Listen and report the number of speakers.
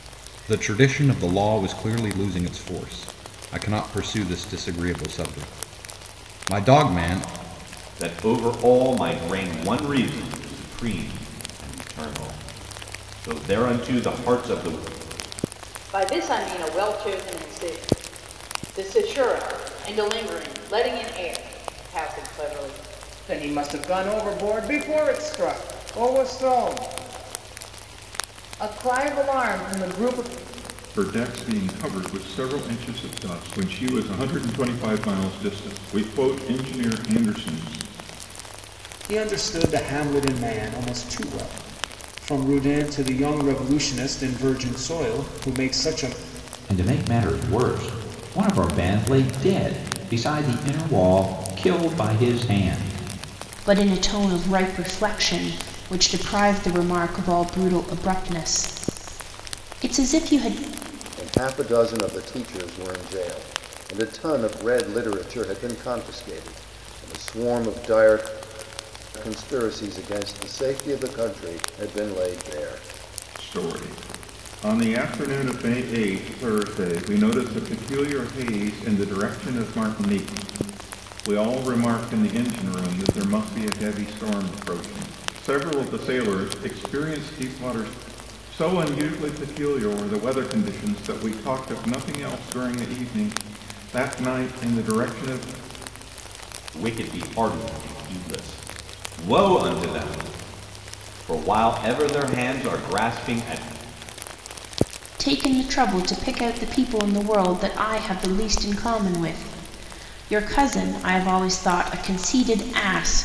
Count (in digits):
9